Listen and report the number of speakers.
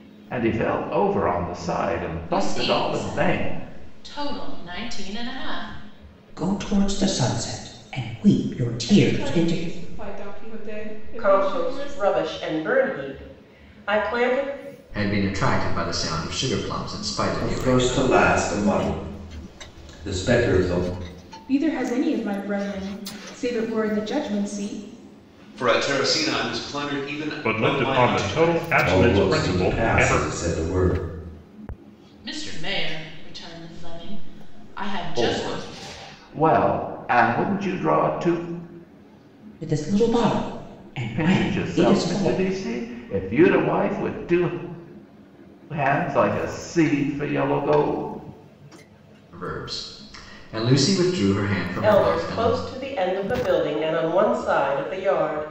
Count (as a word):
ten